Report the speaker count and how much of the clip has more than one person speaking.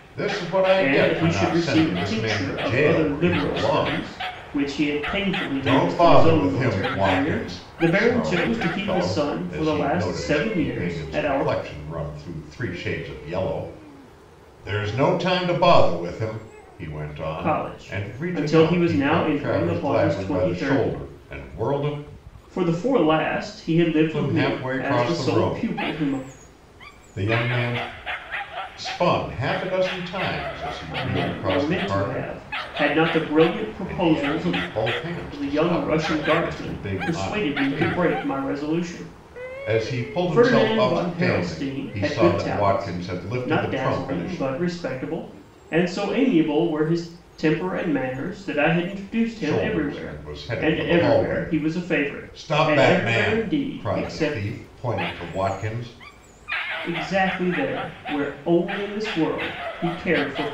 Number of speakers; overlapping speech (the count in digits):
2, about 49%